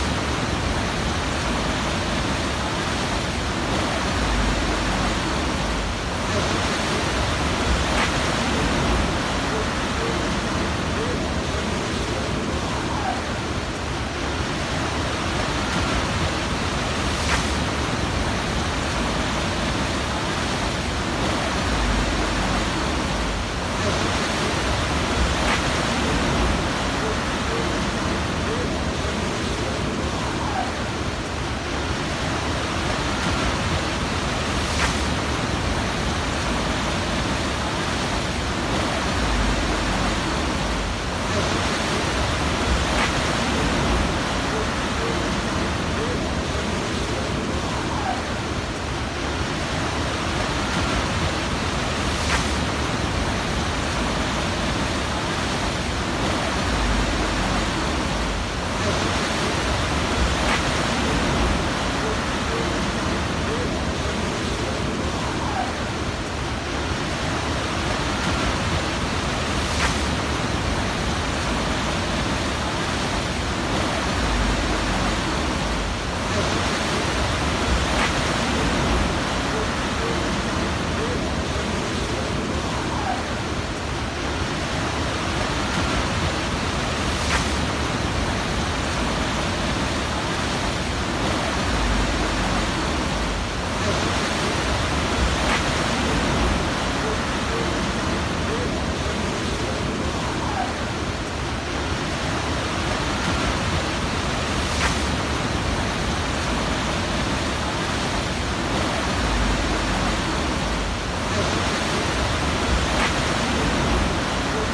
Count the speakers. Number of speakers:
0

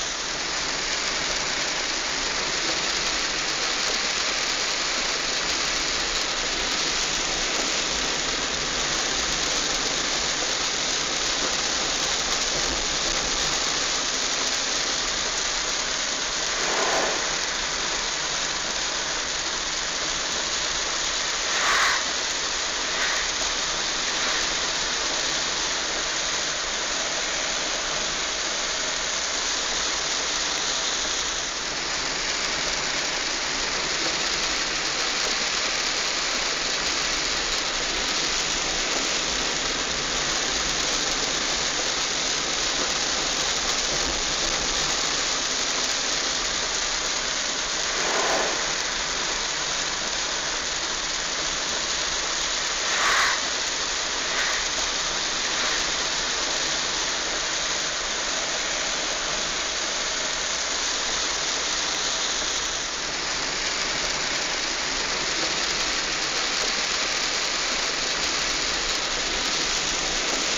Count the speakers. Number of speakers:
0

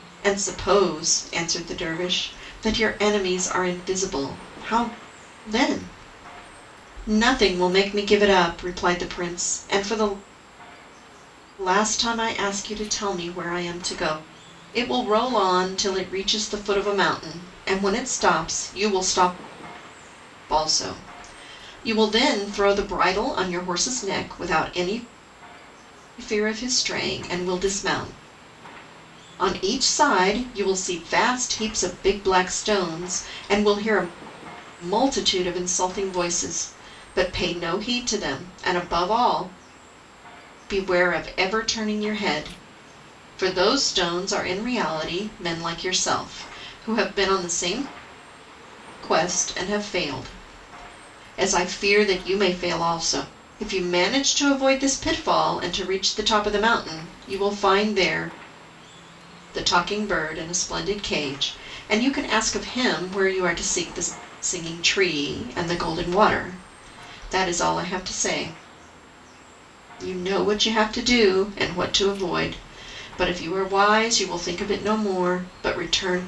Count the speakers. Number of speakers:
1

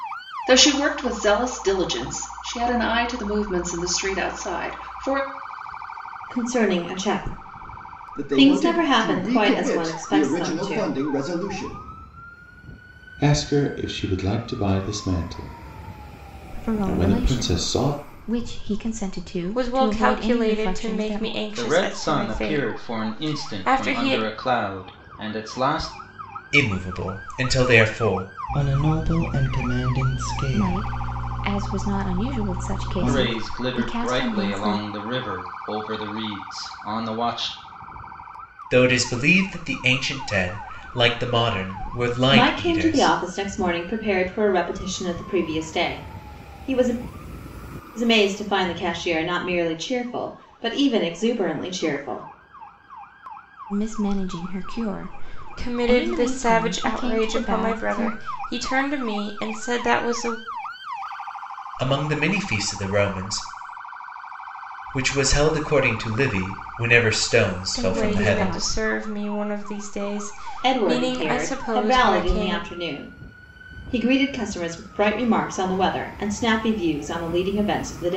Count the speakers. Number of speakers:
9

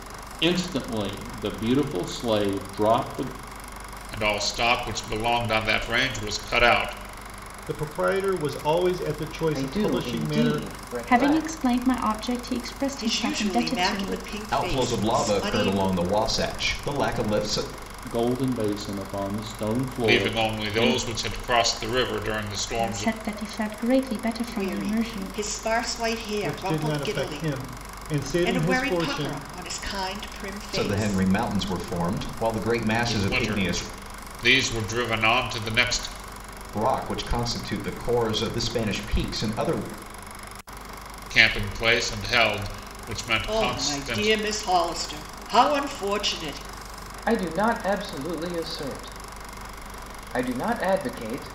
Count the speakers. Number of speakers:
7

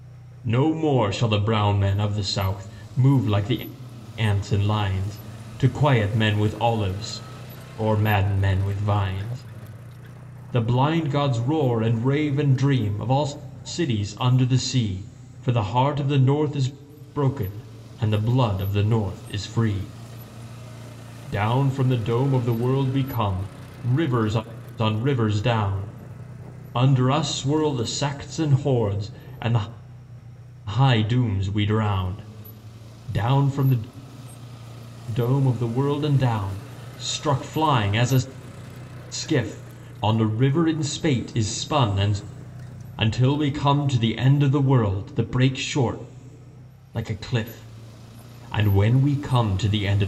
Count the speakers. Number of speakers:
1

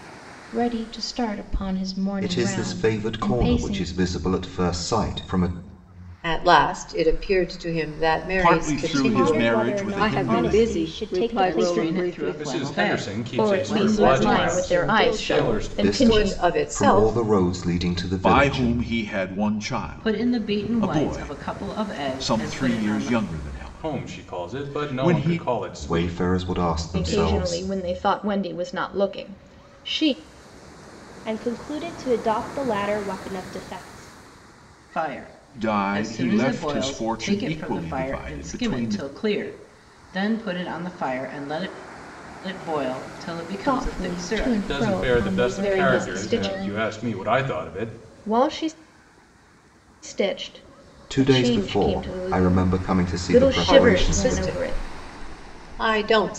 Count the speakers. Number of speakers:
9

